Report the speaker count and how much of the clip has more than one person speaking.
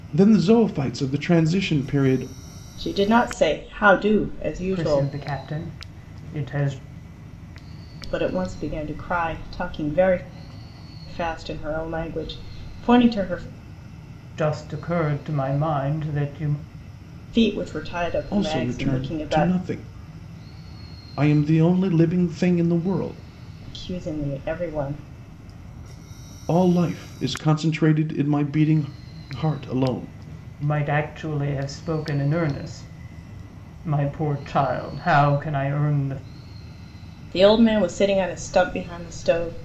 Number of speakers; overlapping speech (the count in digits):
3, about 4%